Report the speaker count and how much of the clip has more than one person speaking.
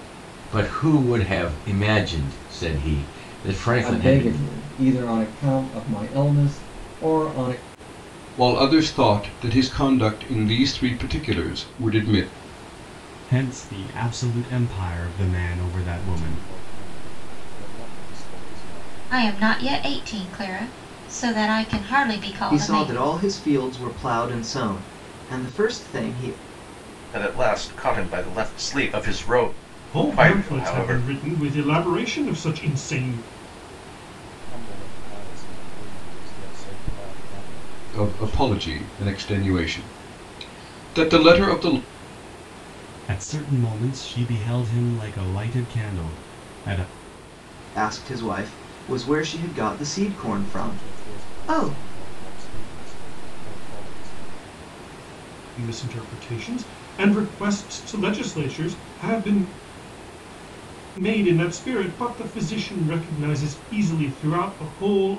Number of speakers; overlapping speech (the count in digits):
9, about 9%